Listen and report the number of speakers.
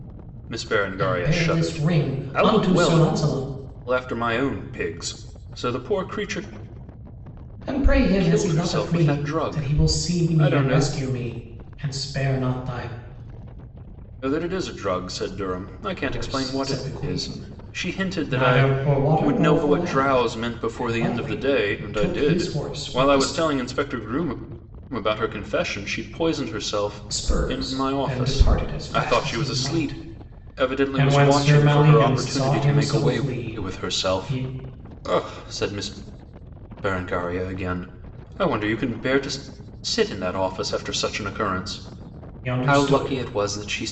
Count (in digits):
2